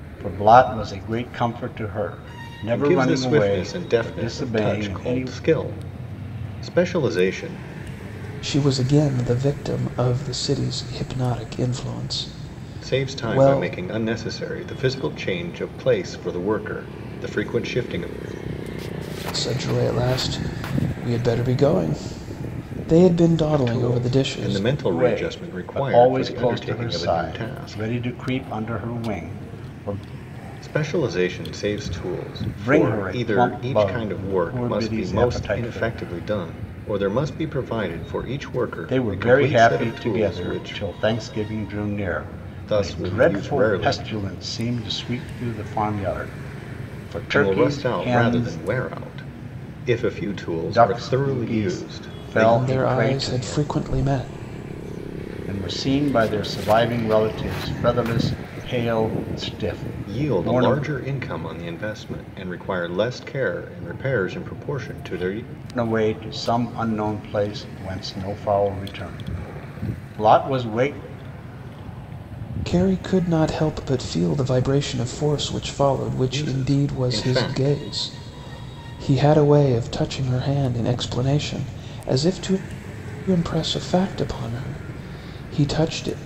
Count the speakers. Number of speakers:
three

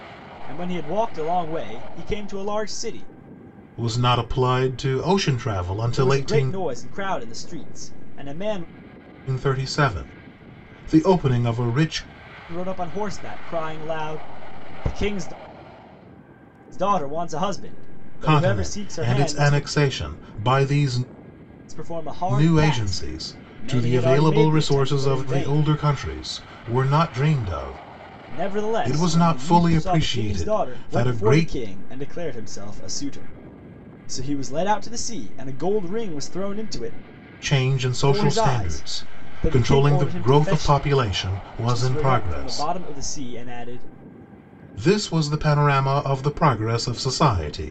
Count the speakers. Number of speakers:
two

